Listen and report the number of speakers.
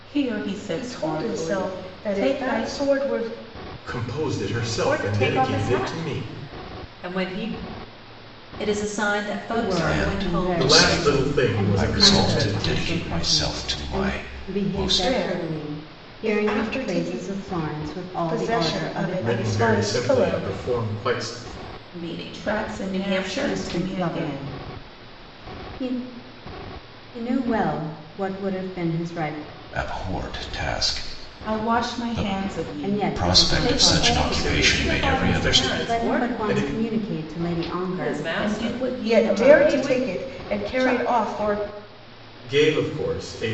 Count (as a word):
seven